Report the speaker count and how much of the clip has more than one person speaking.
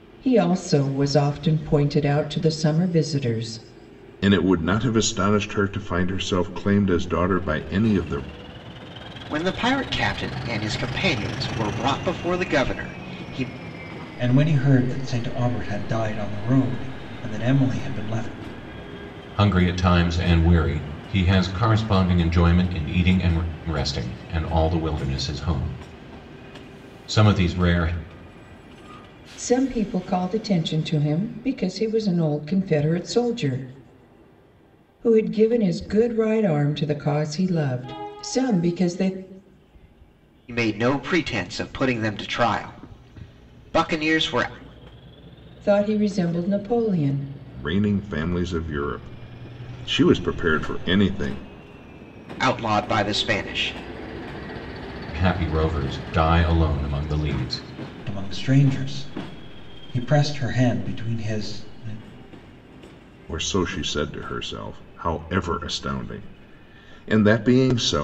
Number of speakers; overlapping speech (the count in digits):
5, no overlap